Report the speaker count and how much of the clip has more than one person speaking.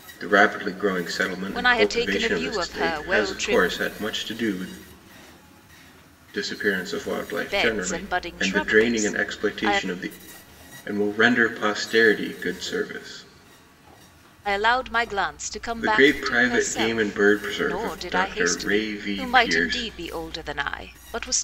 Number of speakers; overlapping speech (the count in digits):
2, about 40%